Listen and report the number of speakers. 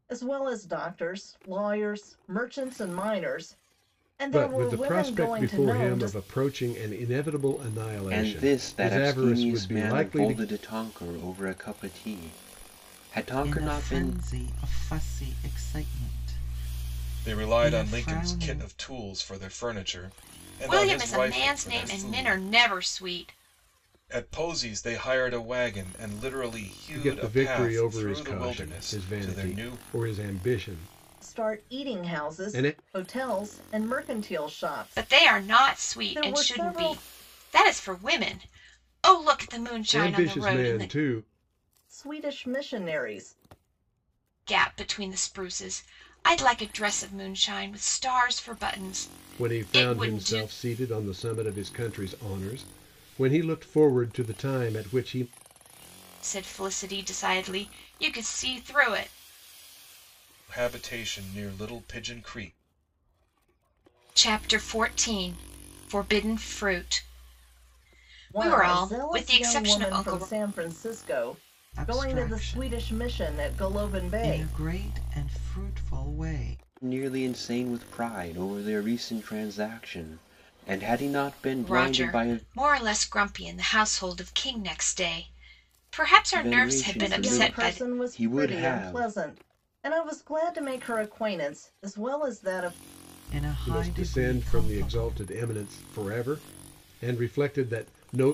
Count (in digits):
6